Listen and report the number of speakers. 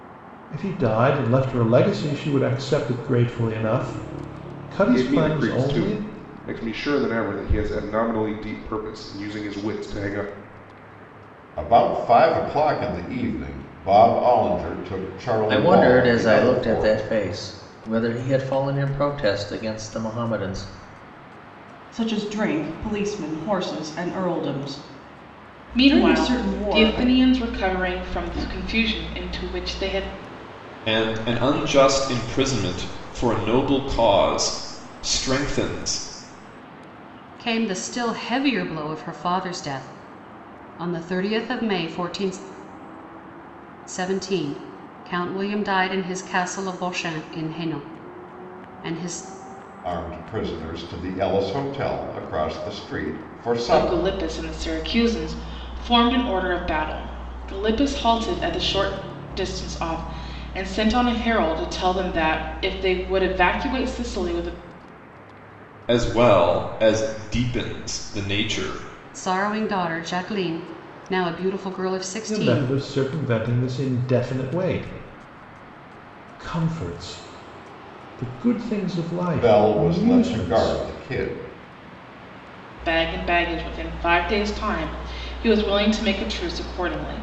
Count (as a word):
eight